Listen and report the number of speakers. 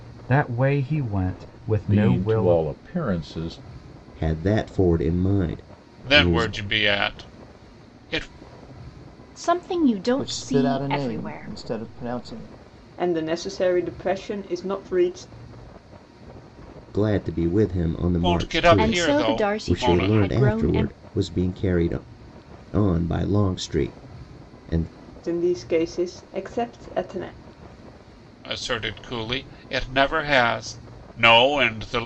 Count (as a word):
seven